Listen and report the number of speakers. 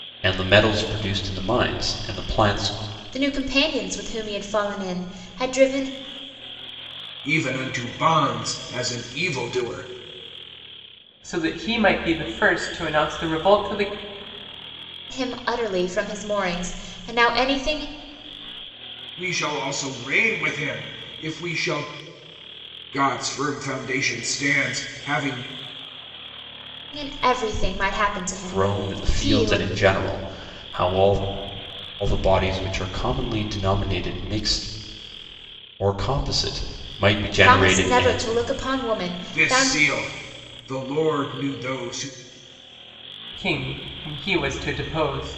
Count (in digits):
4